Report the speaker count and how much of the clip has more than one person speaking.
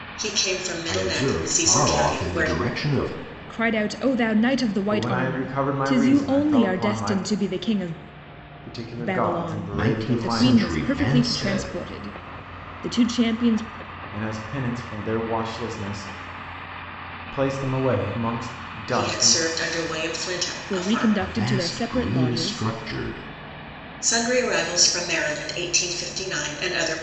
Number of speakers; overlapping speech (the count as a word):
four, about 34%